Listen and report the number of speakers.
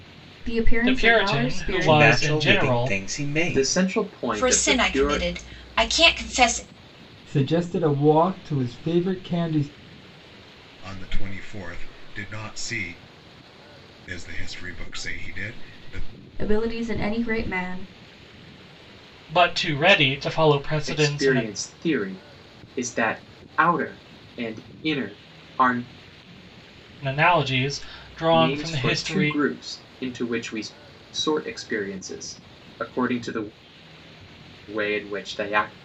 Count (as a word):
seven